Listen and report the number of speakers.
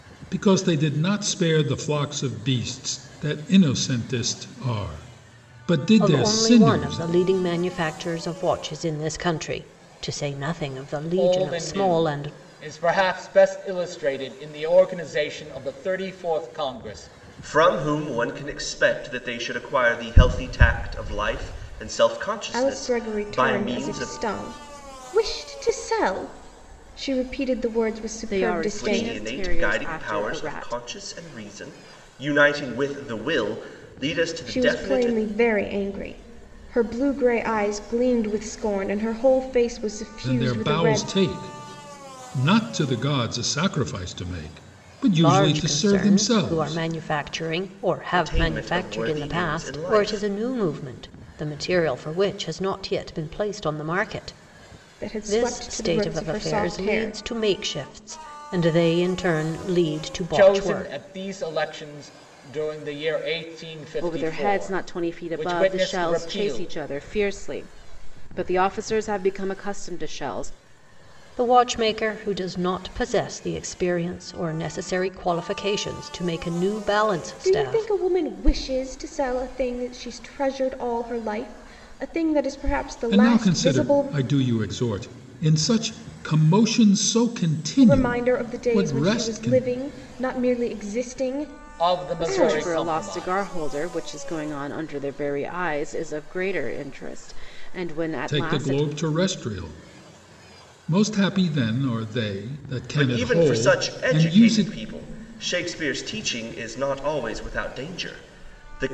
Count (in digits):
6